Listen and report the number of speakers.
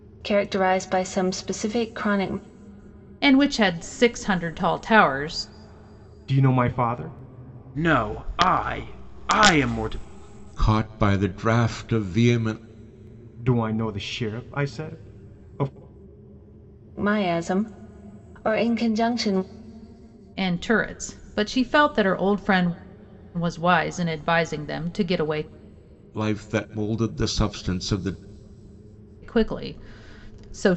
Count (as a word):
five